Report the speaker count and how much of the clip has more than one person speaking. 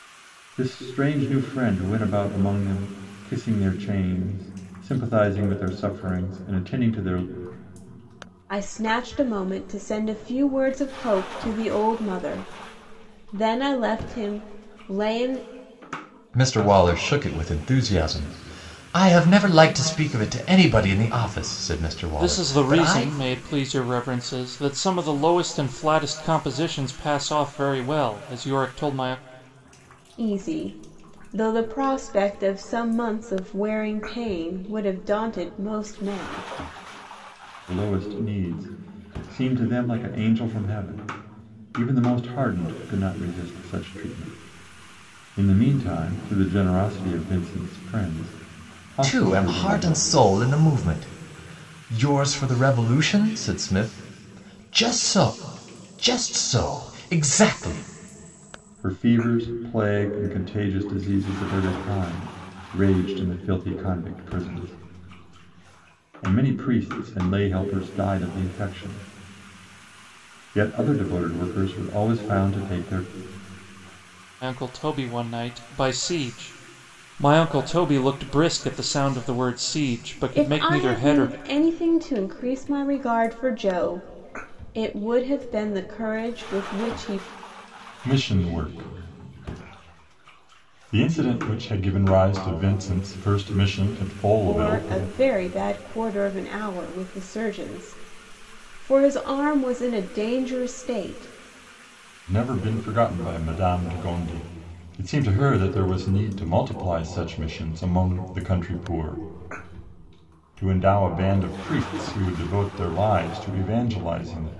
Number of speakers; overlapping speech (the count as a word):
four, about 3%